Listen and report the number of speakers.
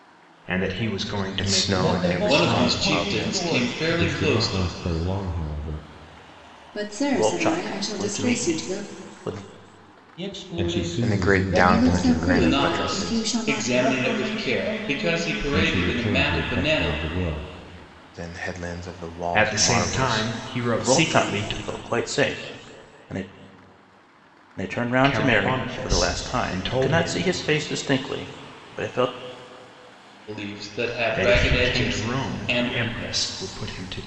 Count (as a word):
seven